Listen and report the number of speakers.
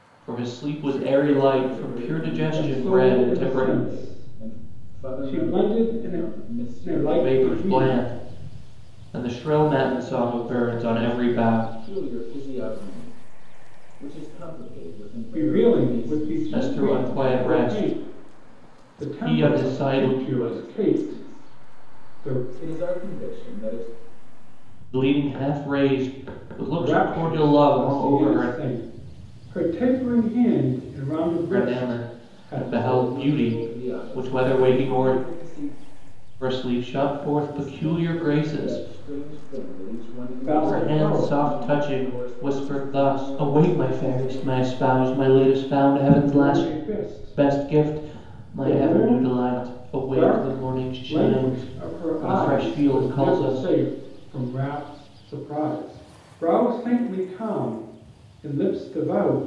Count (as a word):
three